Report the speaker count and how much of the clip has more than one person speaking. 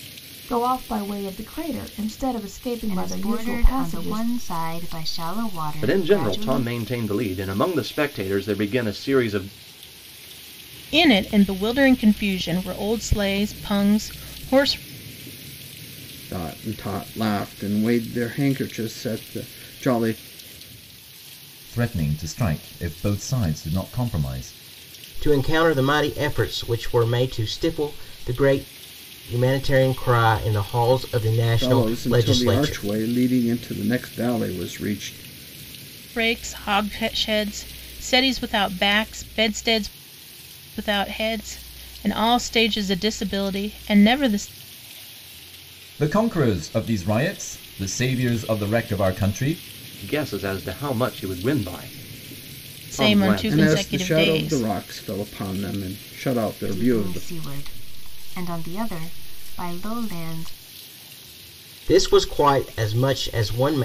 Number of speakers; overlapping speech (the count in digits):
7, about 10%